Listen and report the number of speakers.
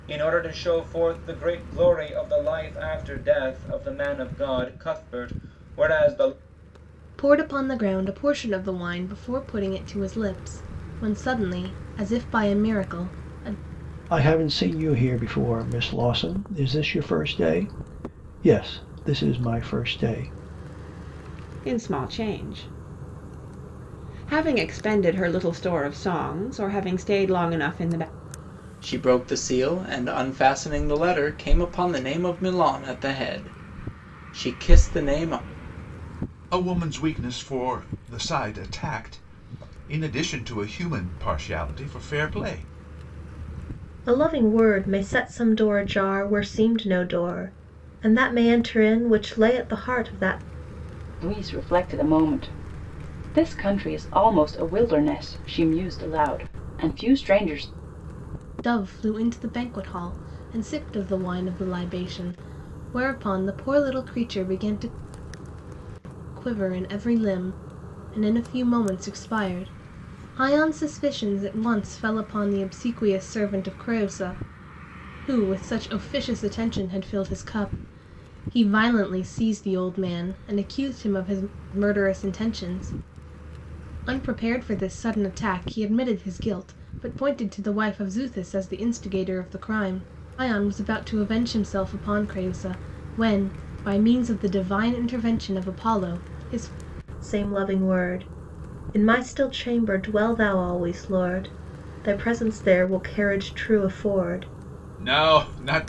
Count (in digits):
8